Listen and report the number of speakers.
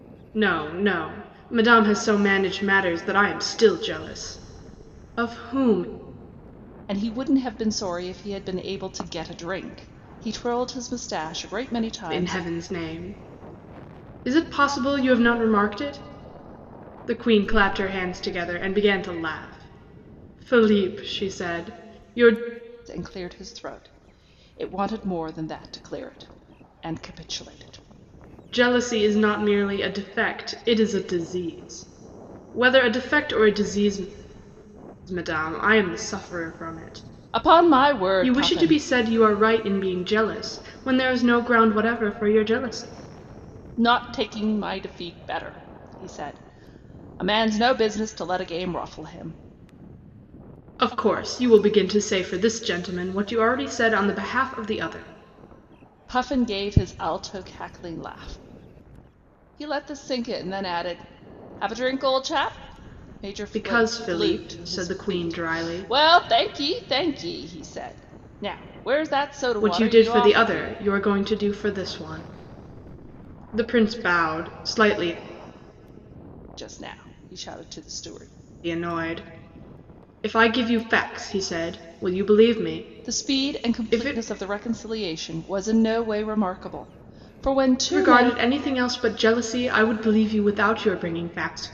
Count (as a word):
two